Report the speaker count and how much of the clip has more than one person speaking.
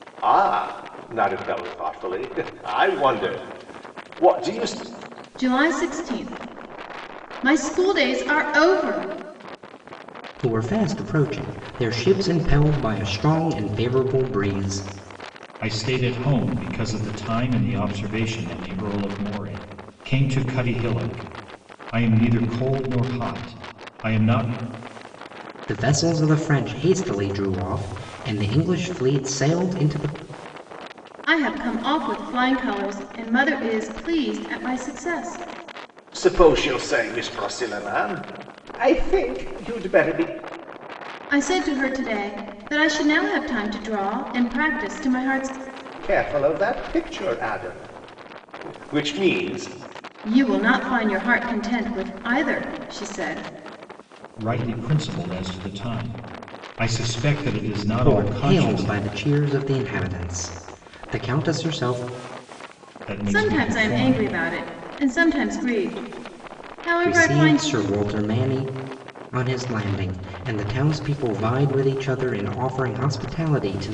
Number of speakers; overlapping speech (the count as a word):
four, about 4%